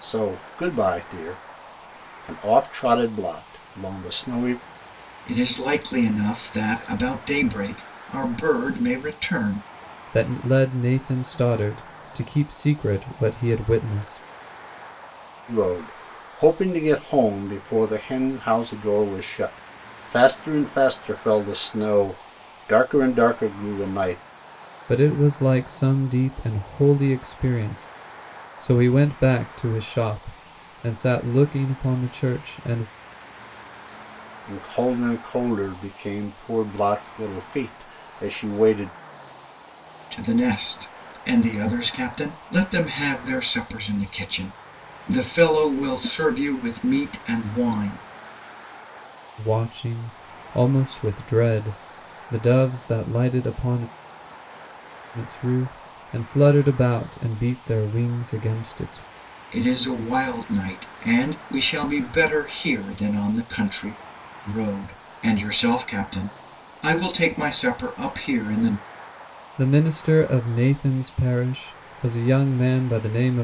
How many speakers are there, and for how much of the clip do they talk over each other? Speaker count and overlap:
three, no overlap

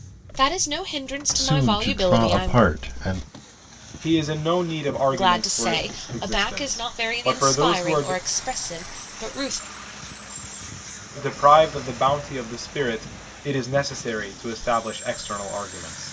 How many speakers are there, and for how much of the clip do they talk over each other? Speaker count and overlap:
three, about 25%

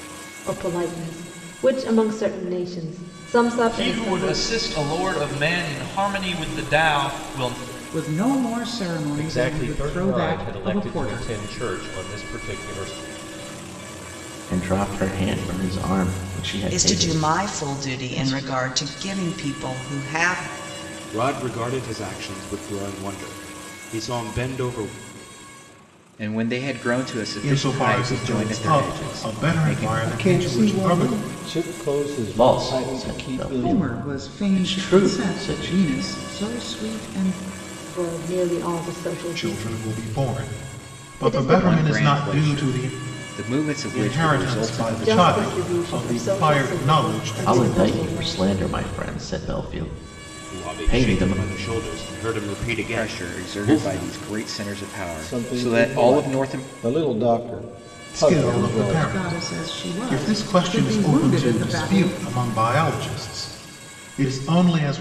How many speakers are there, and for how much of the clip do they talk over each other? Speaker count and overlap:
ten, about 43%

